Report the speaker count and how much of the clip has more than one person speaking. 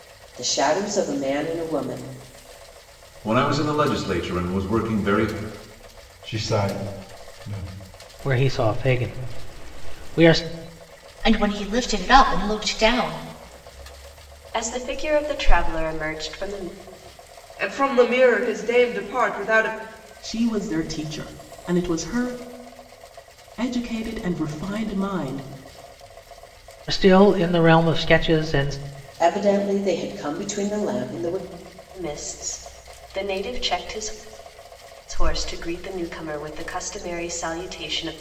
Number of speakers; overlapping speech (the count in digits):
8, no overlap